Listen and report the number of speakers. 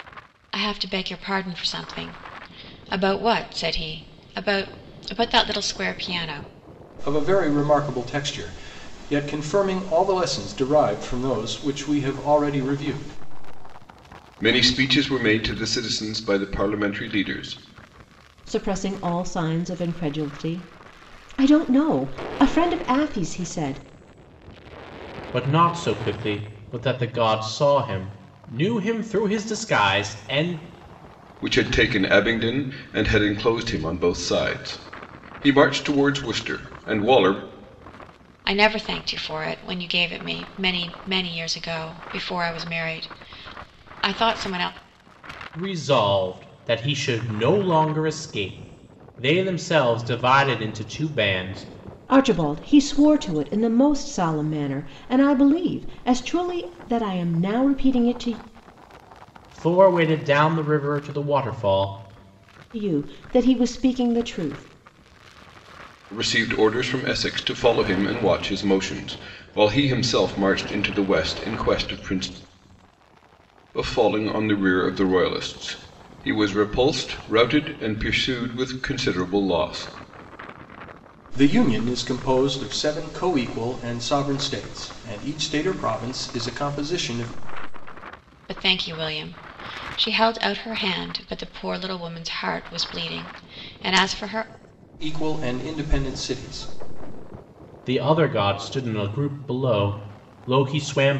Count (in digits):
5